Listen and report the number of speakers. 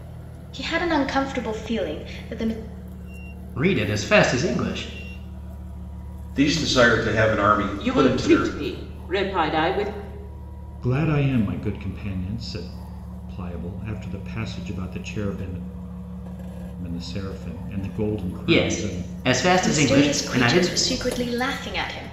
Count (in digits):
5